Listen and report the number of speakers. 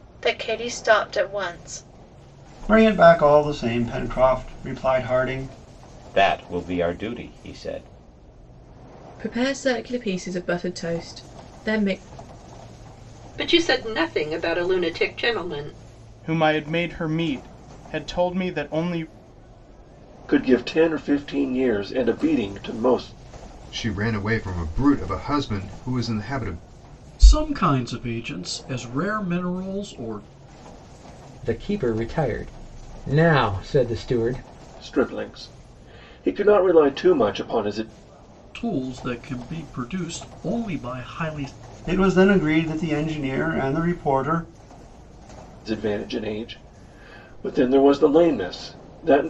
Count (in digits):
10